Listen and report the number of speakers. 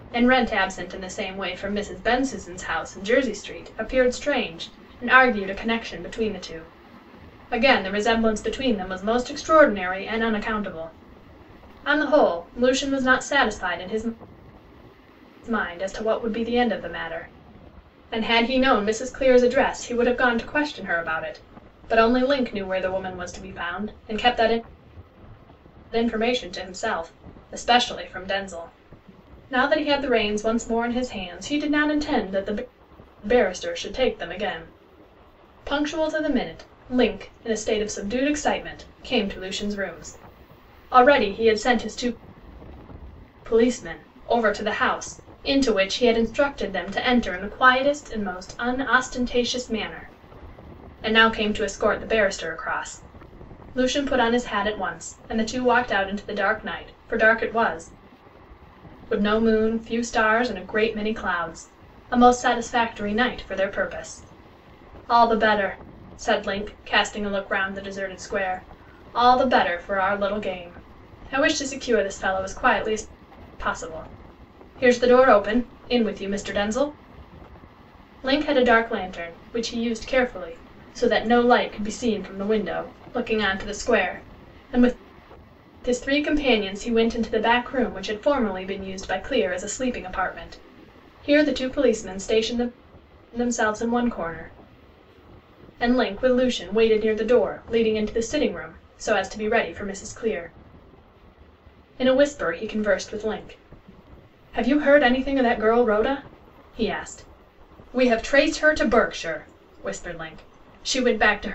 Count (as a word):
one